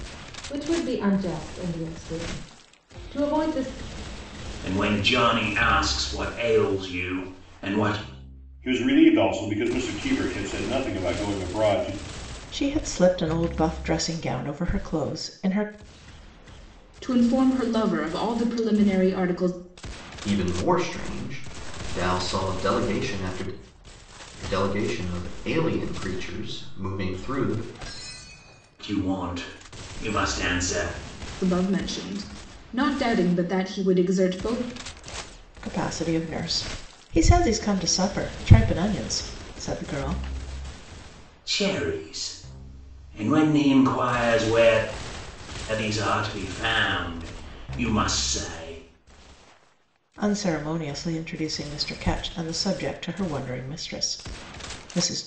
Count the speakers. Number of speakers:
six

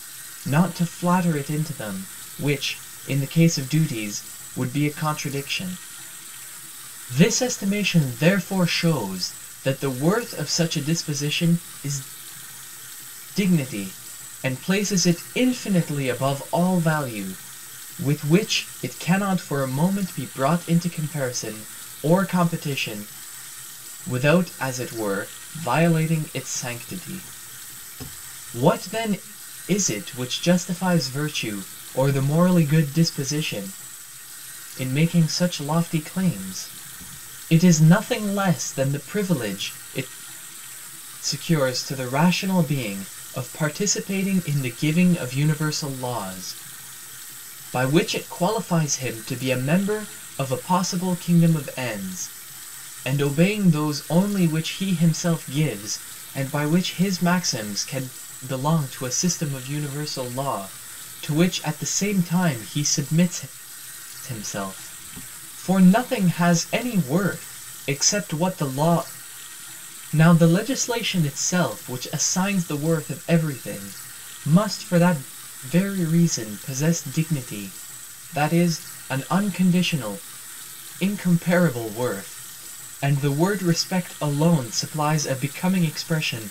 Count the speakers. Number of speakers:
one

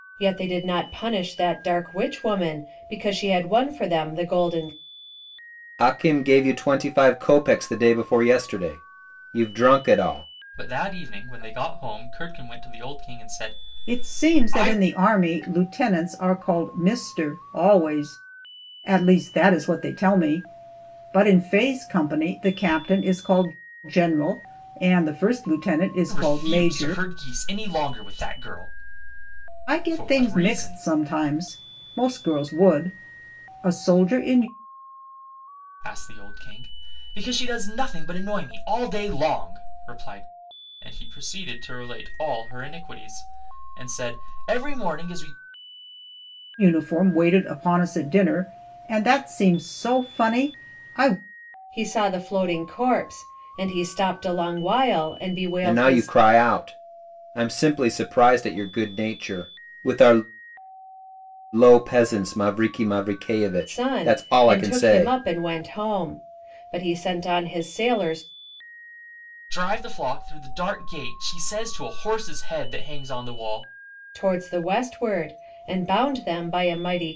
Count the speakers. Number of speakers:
four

